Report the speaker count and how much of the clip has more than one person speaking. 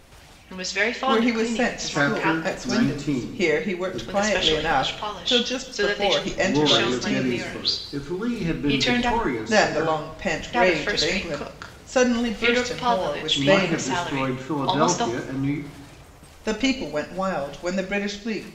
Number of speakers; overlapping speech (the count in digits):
3, about 69%